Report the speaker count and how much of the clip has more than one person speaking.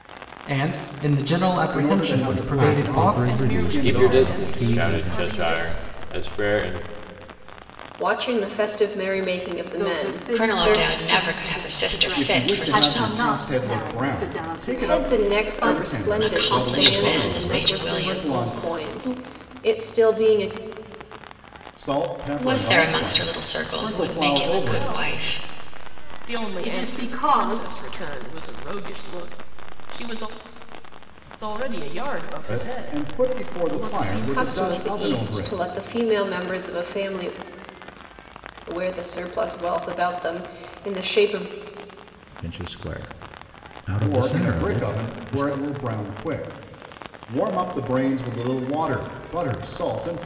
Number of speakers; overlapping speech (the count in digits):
8, about 45%